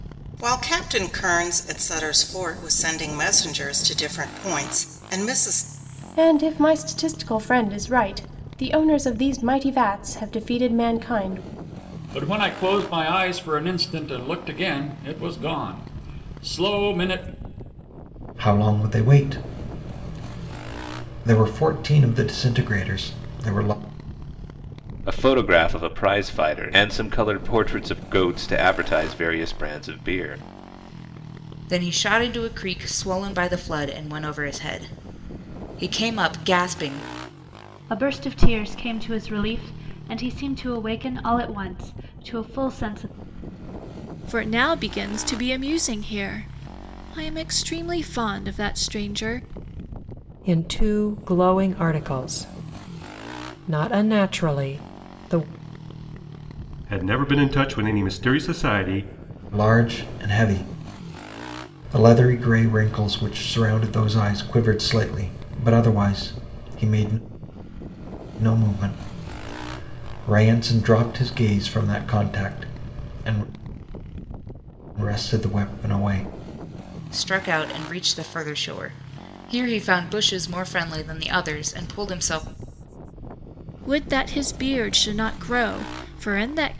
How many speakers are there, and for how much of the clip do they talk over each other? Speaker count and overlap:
ten, no overlap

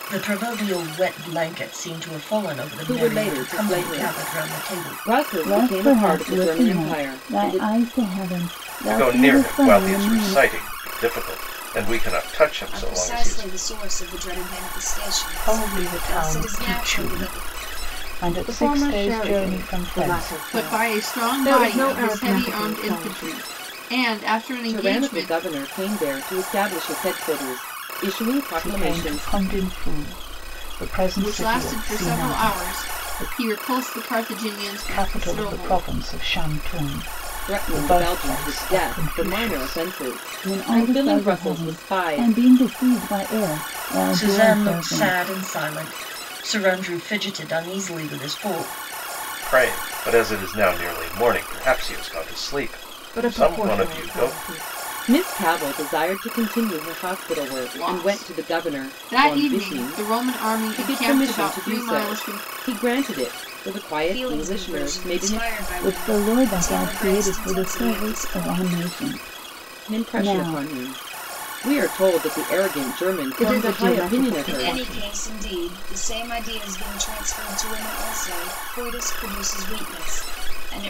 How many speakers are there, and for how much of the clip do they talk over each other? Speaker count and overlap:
eight, about 45%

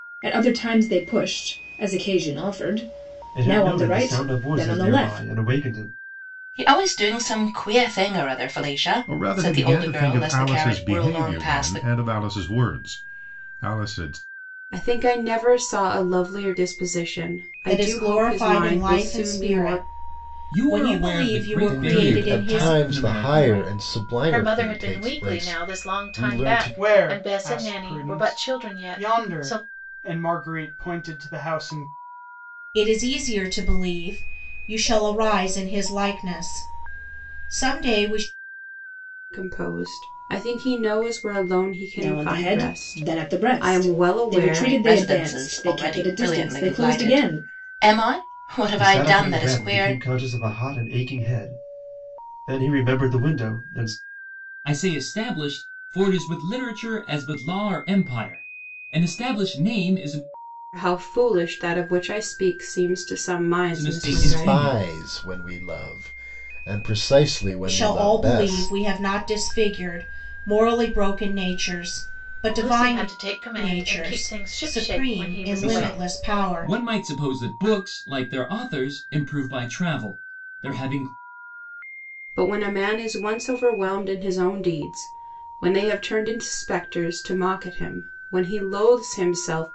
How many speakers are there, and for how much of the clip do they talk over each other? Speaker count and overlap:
ten, about 32%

